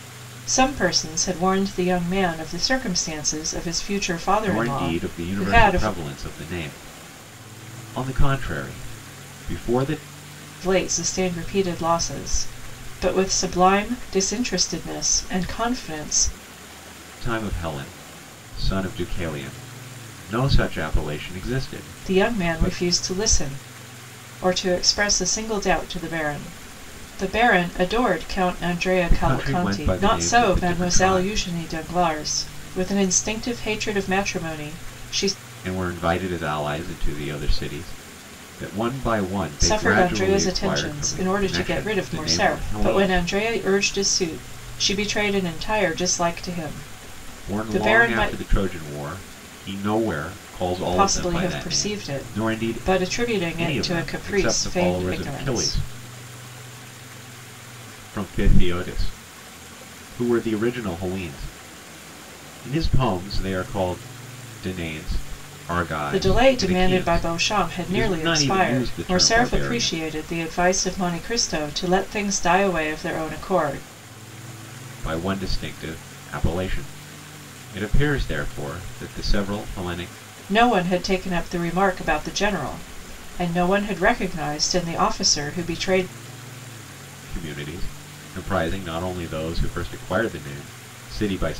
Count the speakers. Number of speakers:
two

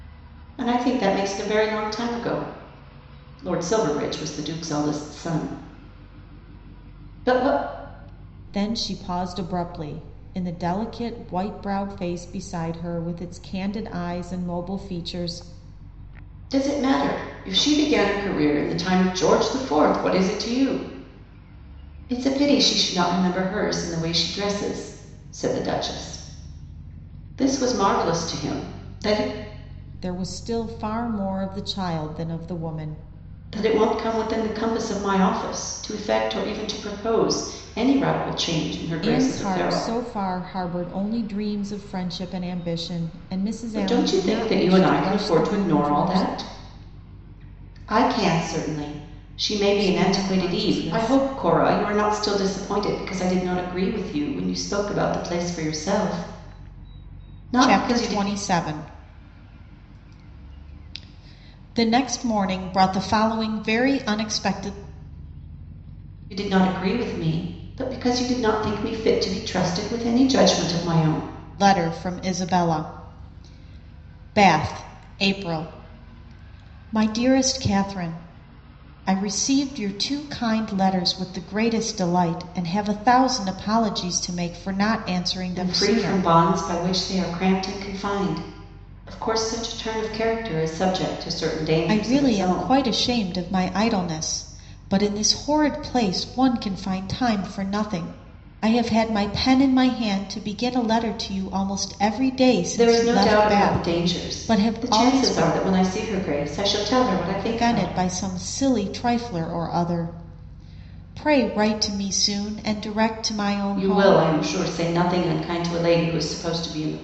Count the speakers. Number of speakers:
two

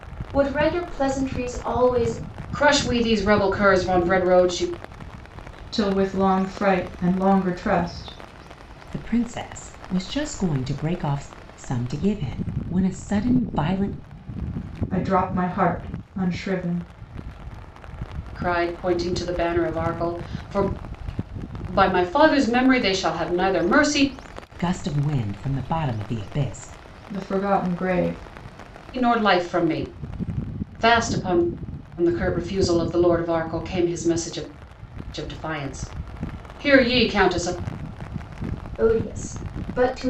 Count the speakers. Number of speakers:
four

